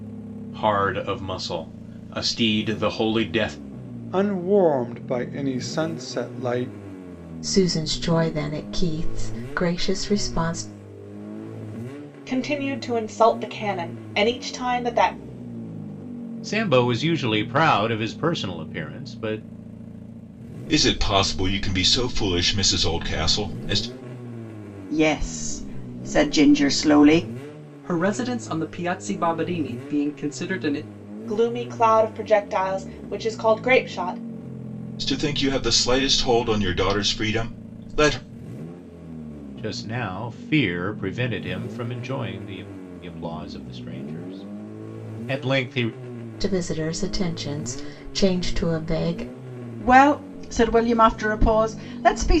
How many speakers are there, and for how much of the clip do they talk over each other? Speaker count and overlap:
8, no overlap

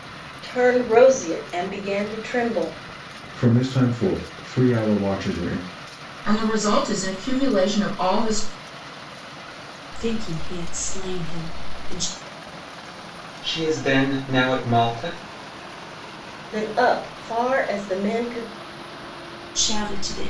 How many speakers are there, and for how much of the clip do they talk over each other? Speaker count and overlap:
5, no overlap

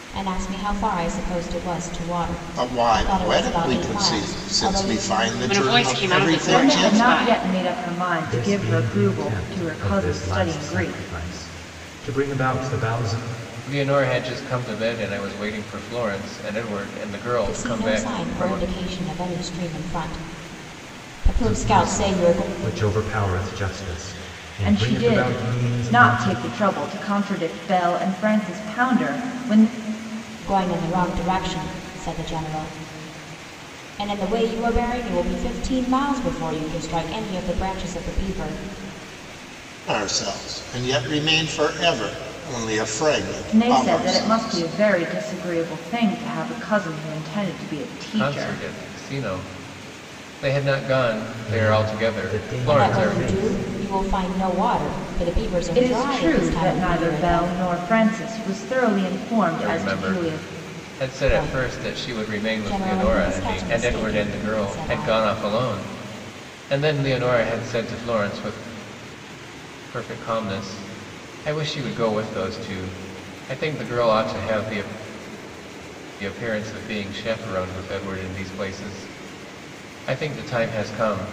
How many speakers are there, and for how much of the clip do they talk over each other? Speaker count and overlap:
6, about 27%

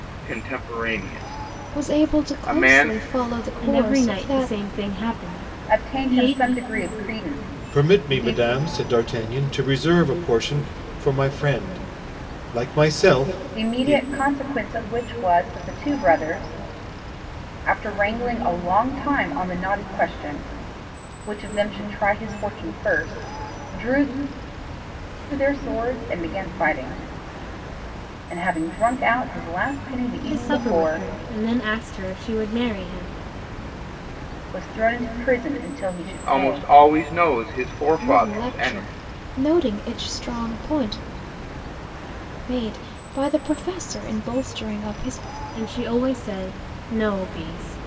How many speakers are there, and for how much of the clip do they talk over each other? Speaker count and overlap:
5, about 13%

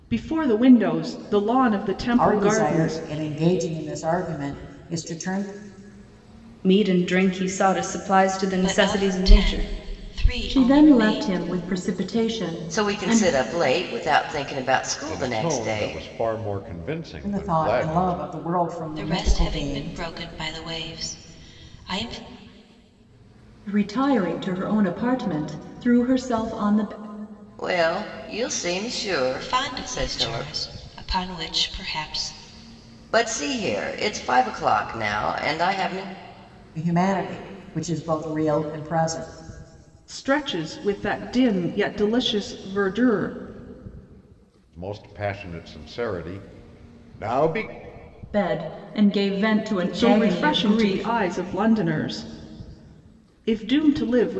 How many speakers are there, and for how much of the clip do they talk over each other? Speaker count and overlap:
7, about 17%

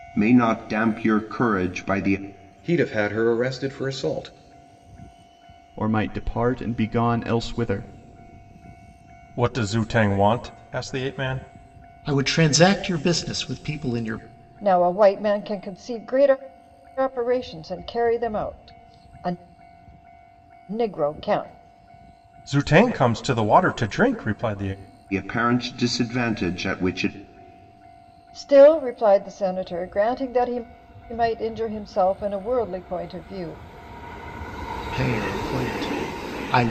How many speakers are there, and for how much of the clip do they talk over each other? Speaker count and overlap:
6, no overlap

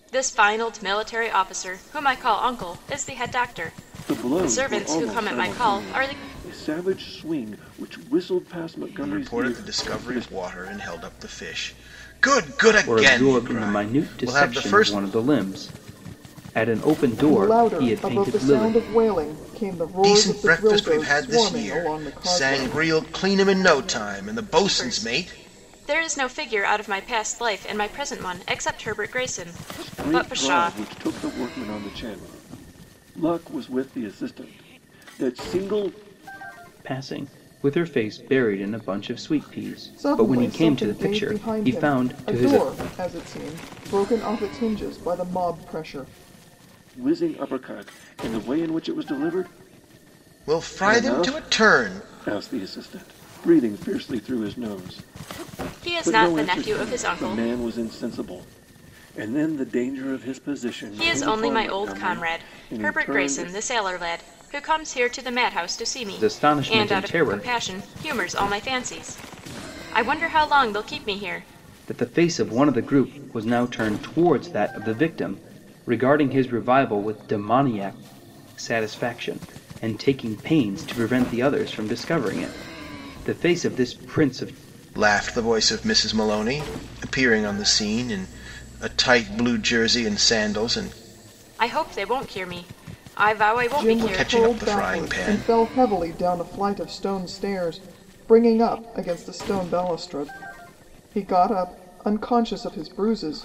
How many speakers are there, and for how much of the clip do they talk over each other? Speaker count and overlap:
5, about 23%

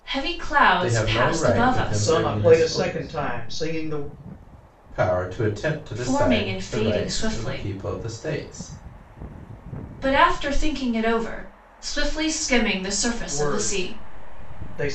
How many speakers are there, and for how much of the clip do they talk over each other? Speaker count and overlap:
4, about 33%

